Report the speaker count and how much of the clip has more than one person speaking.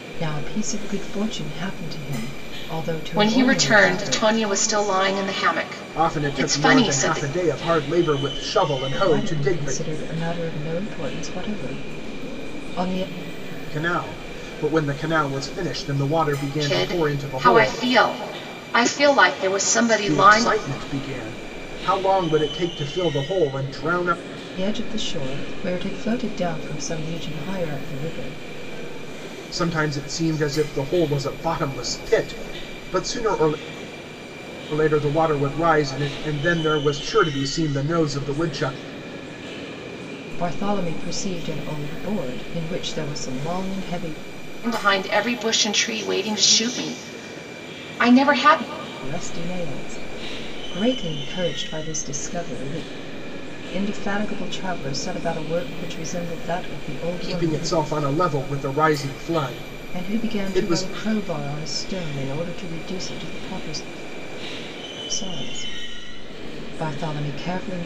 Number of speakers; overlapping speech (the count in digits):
3, about 10%